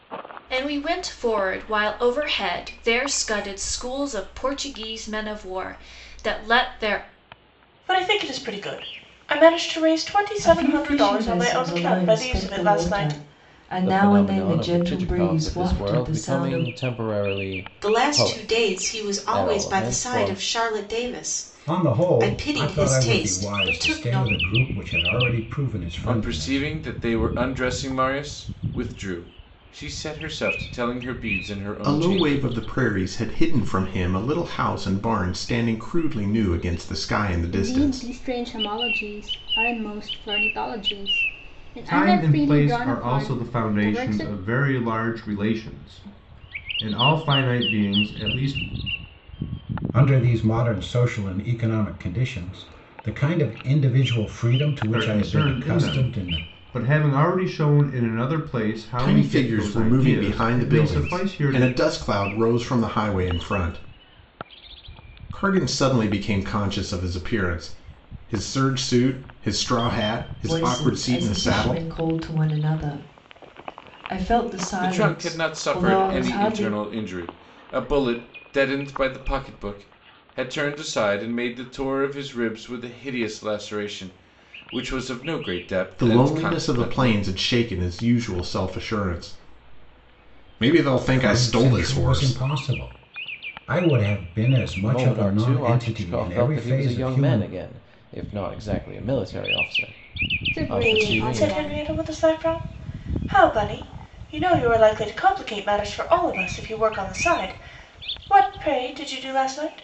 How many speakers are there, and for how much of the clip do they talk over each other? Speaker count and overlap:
ten, about 27%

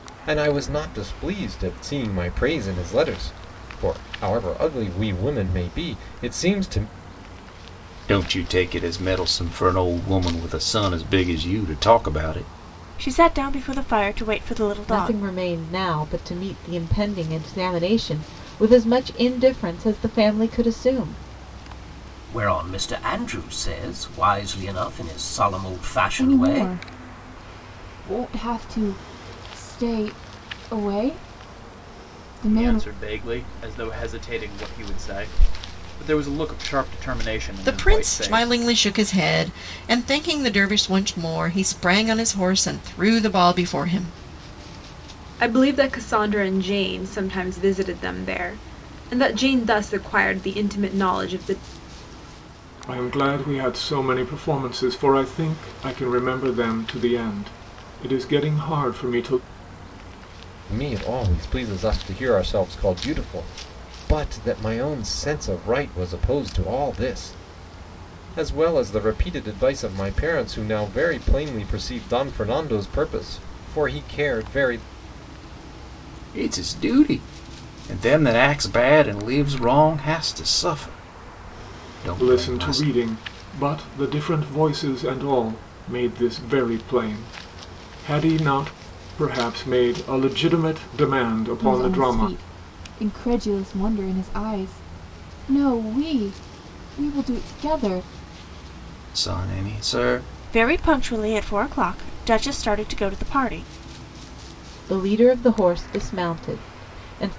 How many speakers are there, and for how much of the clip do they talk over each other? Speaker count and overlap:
ten, about 4%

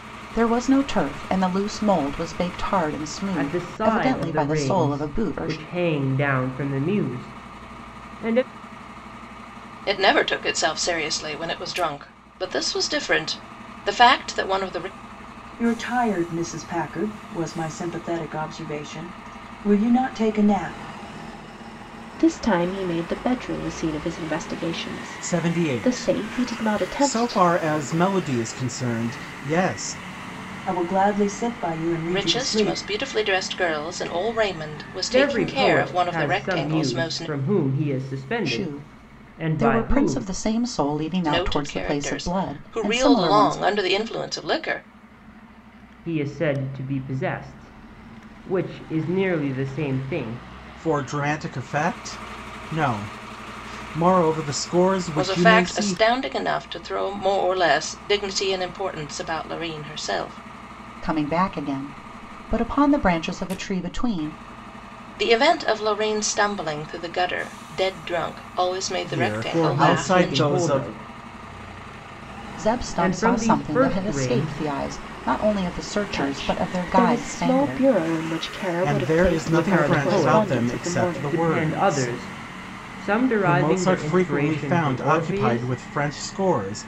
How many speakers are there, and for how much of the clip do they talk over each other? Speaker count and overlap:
six, about 28%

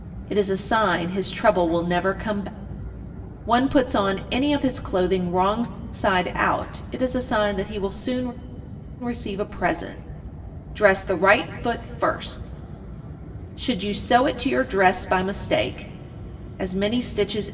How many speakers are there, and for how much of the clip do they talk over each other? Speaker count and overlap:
one, no overlap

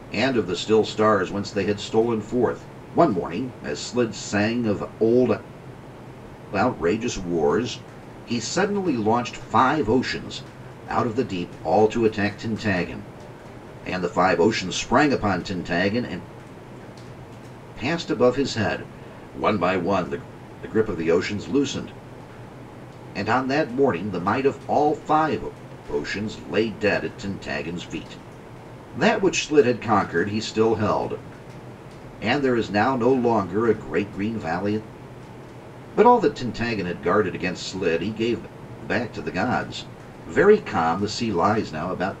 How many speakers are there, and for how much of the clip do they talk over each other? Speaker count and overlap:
one, no overlap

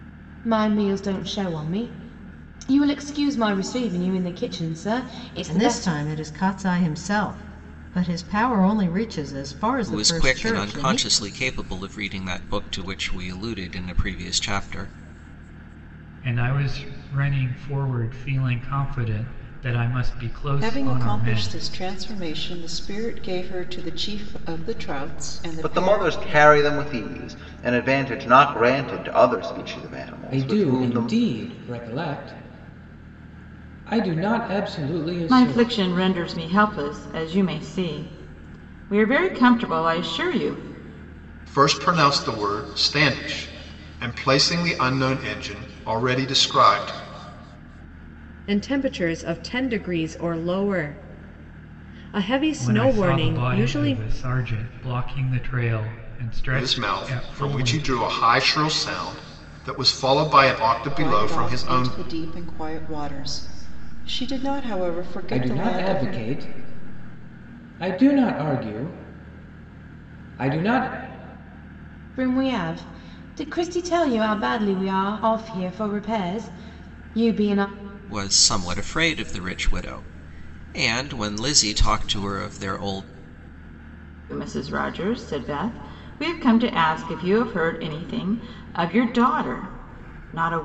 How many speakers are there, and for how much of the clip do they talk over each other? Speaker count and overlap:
ten, about 11%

